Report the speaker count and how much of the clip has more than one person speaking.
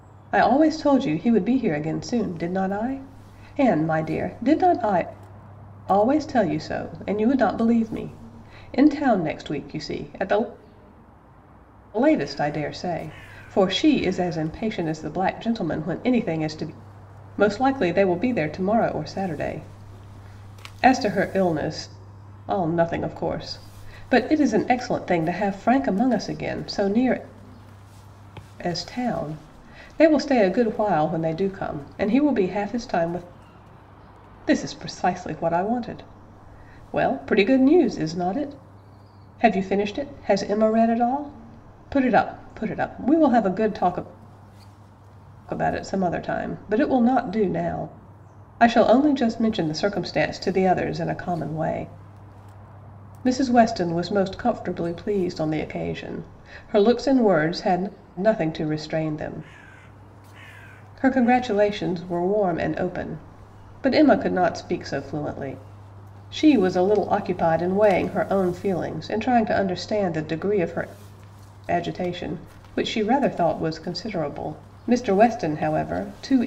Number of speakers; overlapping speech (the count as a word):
one, no overlap